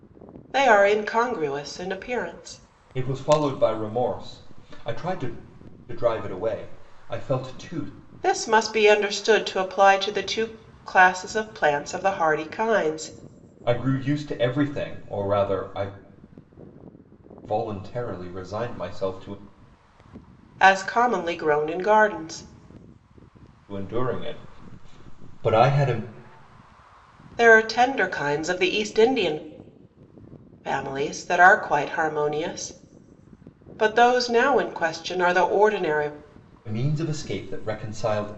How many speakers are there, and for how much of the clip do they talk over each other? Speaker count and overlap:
two, no overlap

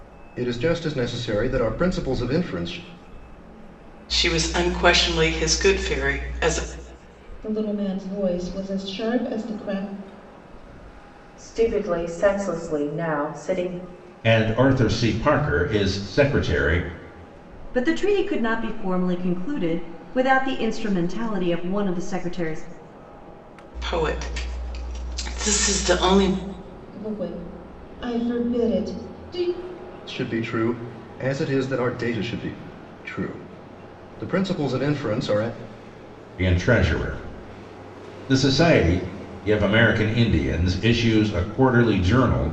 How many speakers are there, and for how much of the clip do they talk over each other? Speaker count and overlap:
six, no overlap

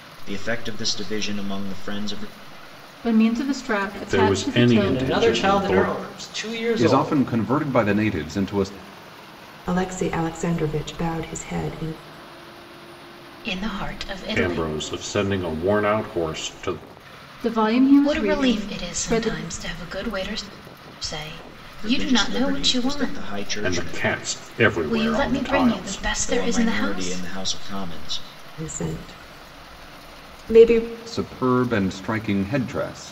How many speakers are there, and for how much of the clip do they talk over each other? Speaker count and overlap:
seven, about 26%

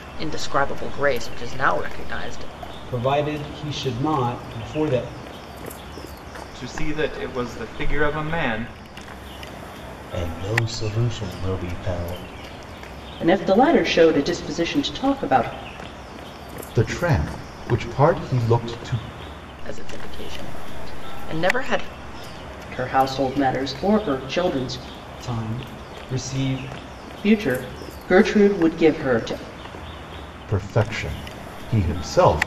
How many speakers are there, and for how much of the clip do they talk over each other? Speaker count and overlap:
six, no overlap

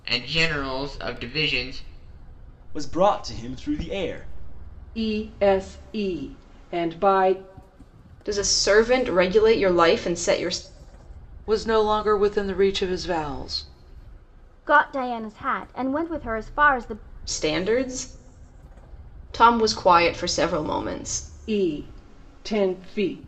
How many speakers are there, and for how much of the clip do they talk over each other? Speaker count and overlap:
six, no overlap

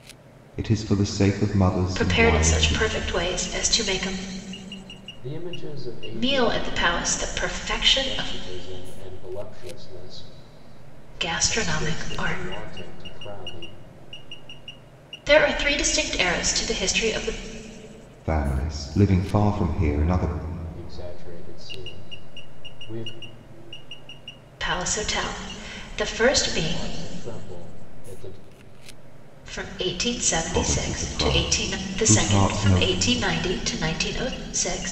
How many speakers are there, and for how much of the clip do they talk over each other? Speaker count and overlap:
three, about 17%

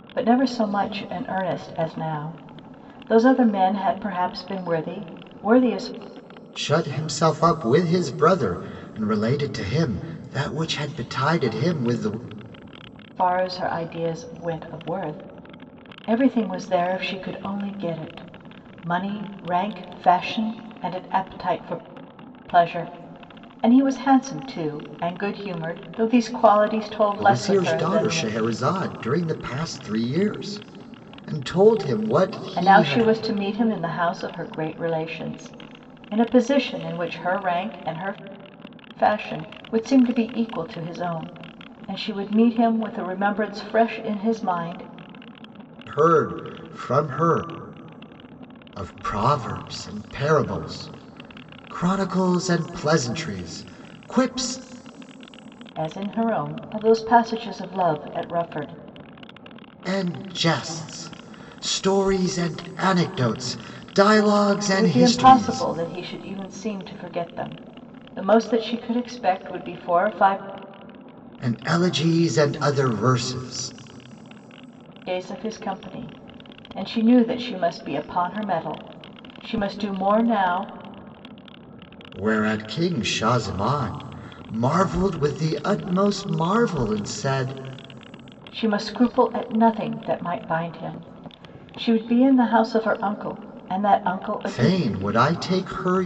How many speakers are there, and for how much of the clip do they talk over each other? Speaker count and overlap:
two, about 3%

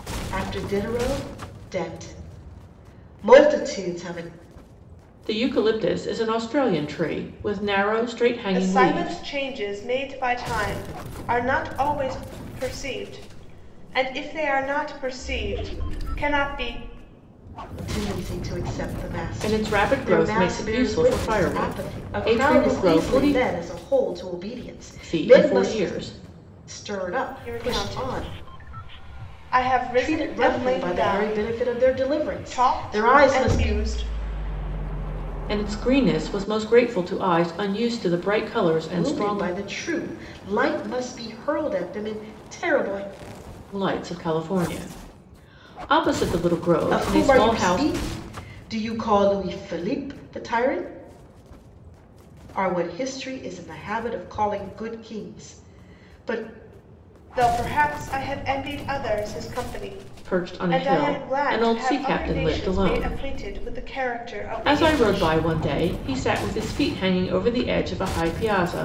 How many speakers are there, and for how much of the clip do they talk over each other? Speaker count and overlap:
three, about 22%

